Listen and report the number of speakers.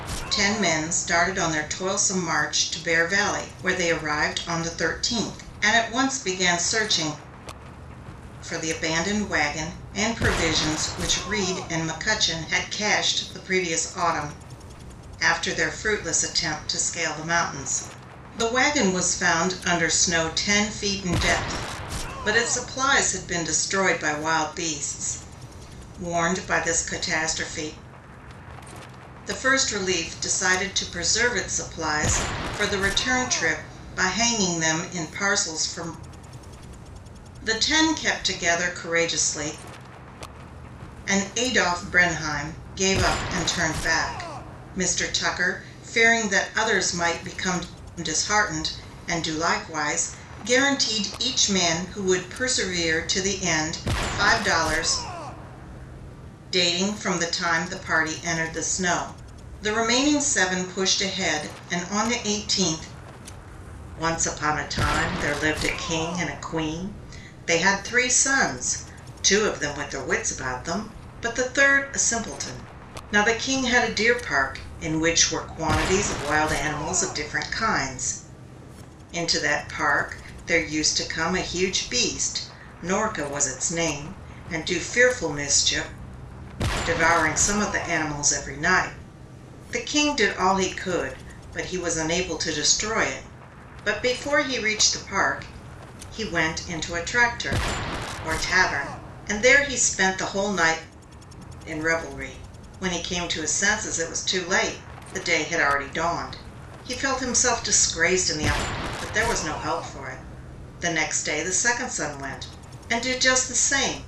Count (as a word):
one